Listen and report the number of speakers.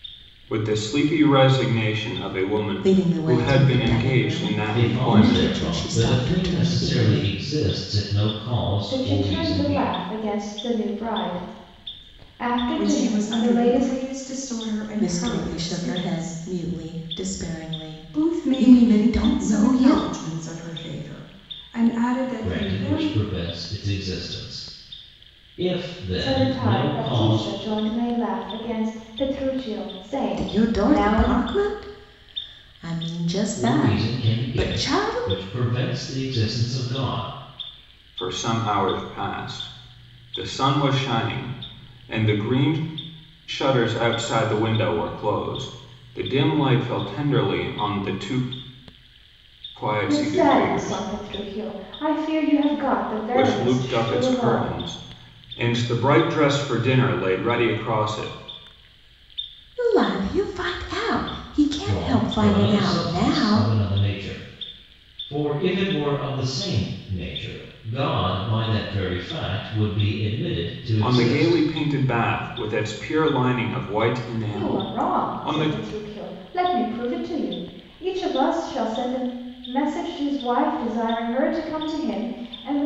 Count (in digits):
5